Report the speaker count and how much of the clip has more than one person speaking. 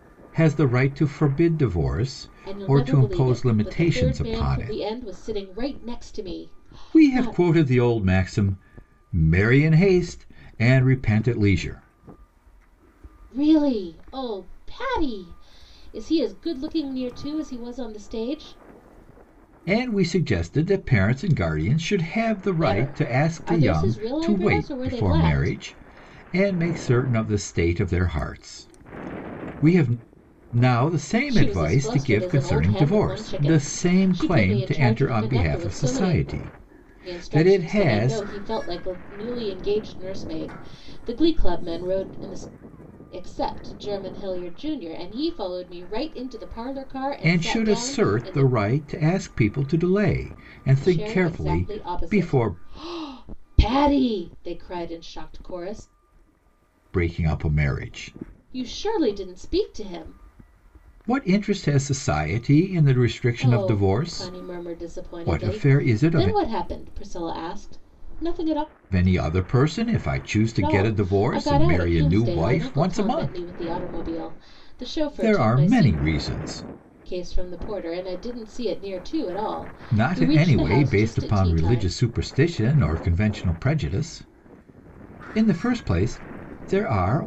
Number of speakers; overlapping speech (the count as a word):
two, about 28%